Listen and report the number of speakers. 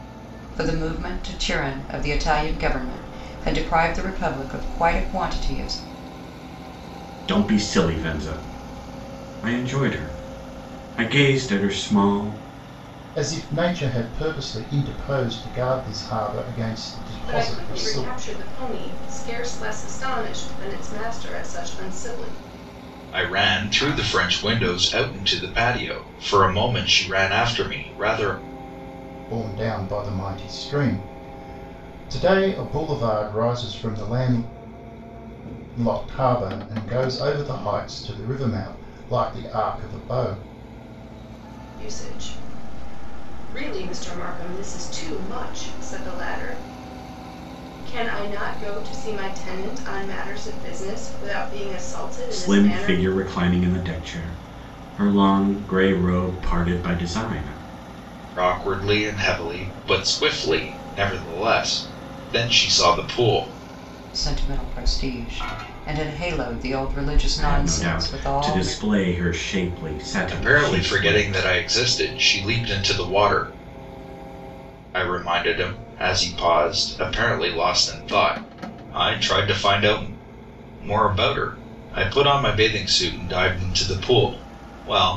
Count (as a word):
five